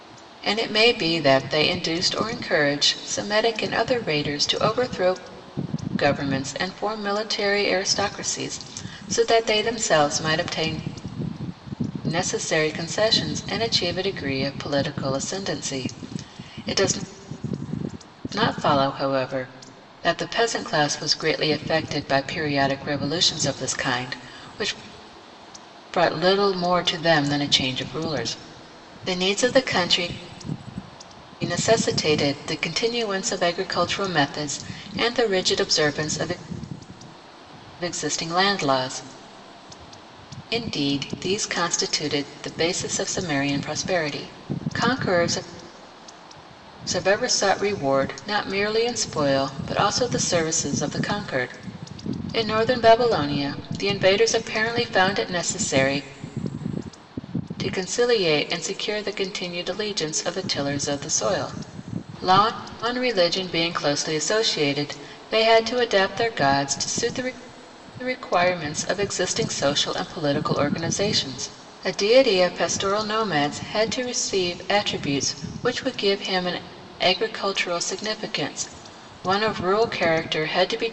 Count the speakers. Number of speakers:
1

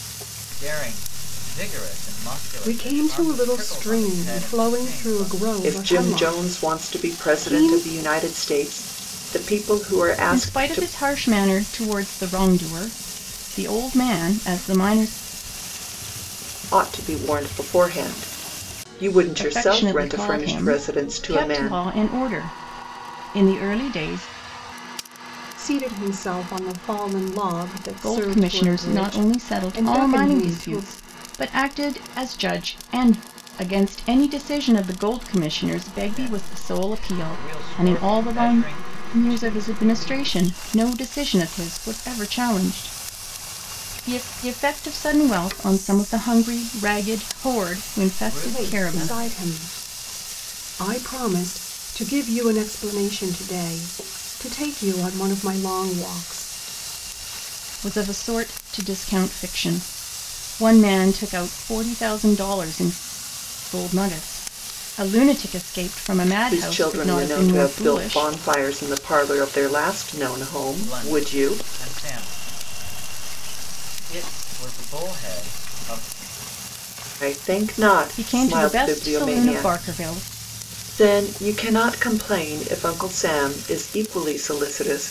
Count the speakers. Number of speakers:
4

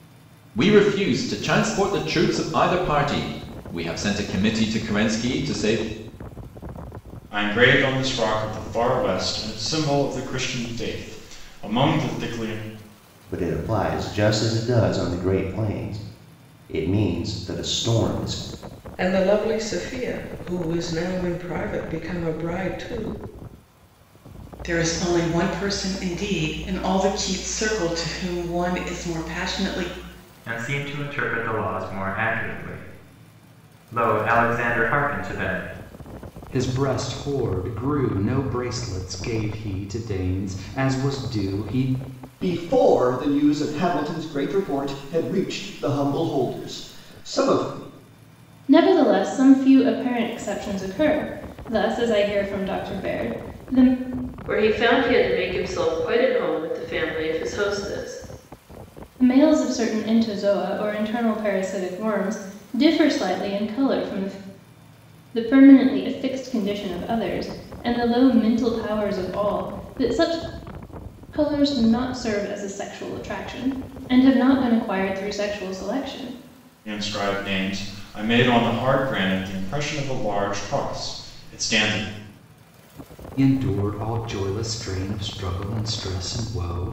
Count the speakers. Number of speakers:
10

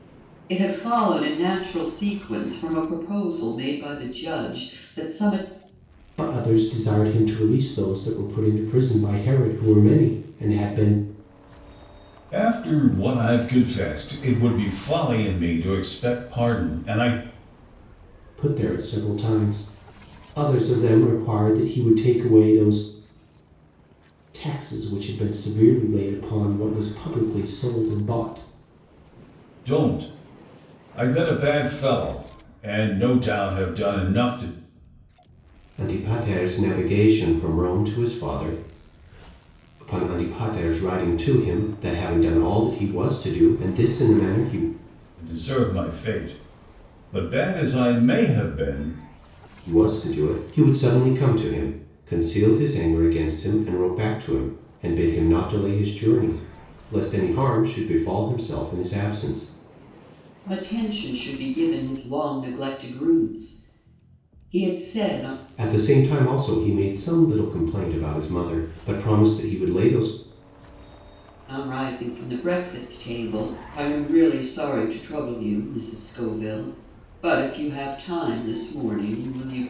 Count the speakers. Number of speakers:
3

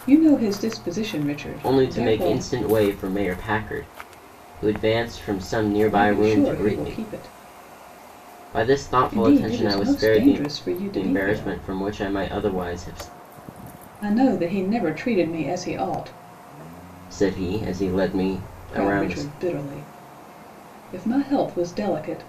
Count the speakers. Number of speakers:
2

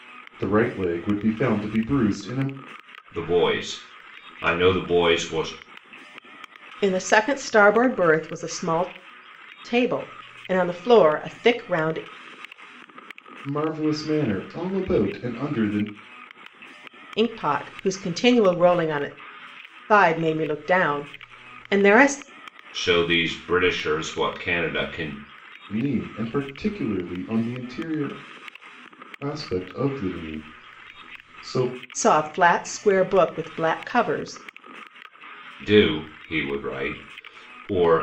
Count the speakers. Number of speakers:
3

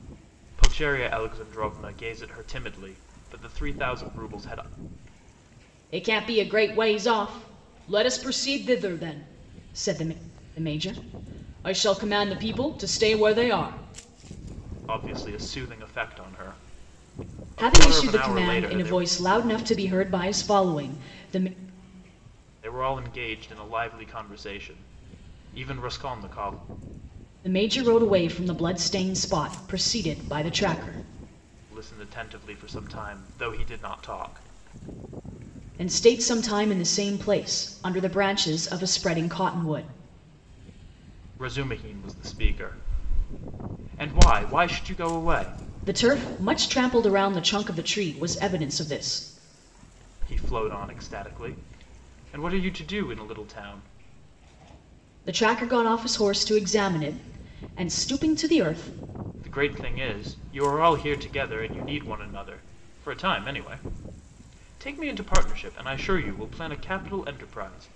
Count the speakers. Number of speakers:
2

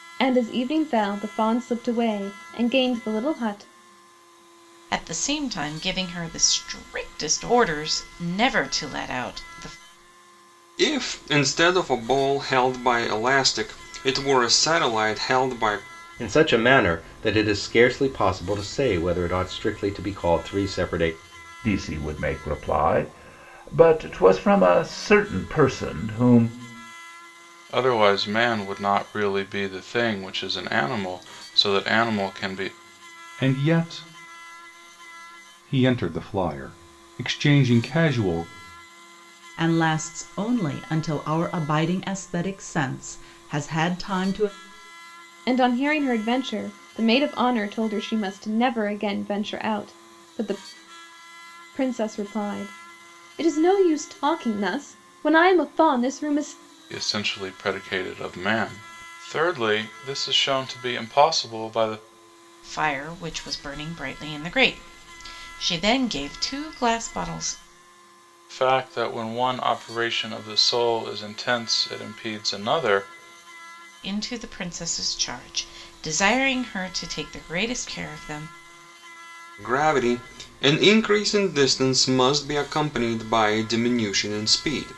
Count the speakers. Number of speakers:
8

